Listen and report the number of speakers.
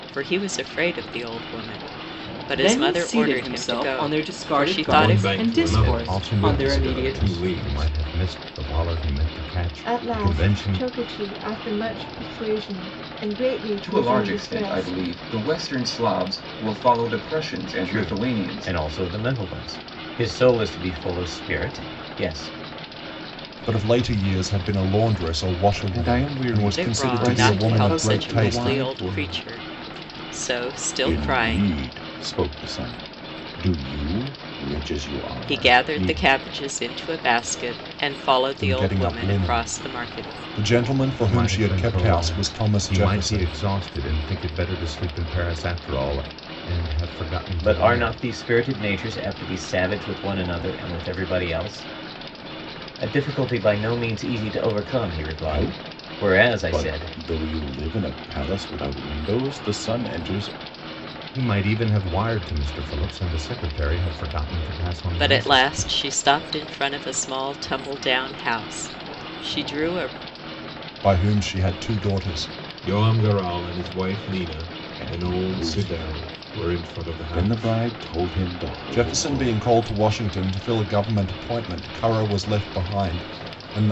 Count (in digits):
9